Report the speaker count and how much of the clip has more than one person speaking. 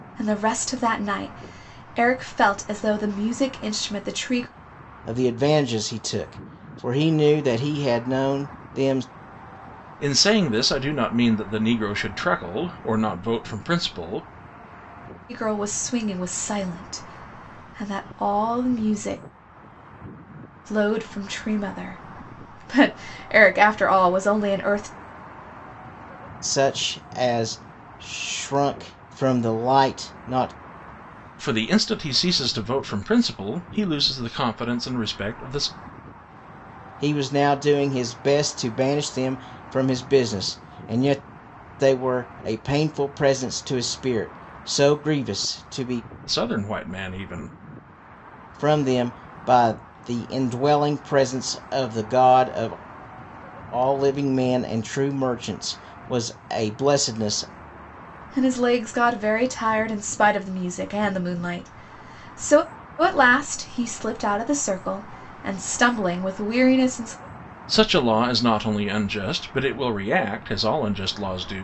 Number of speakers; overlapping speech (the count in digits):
3, no overlap